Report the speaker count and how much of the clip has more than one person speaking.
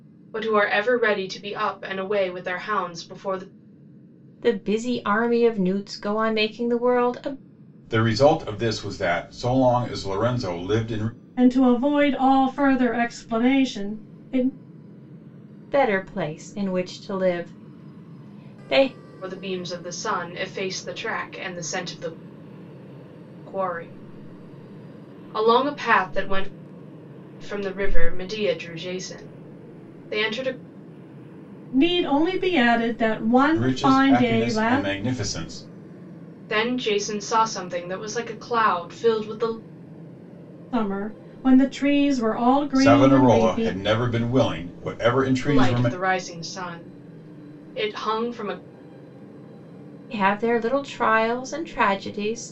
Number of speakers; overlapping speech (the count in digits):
4, about 5%